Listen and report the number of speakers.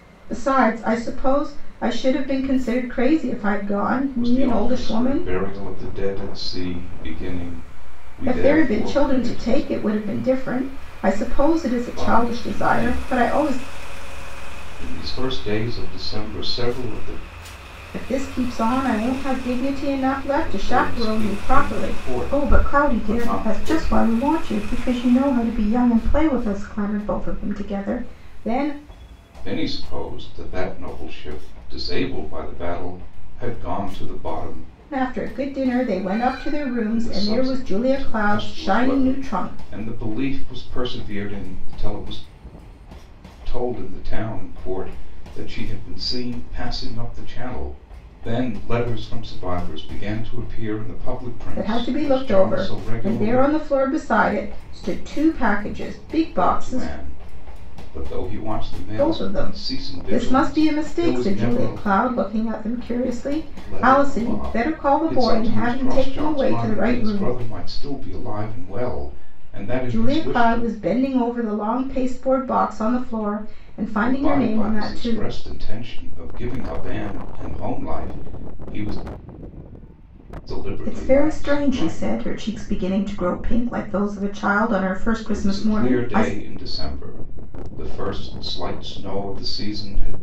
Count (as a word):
two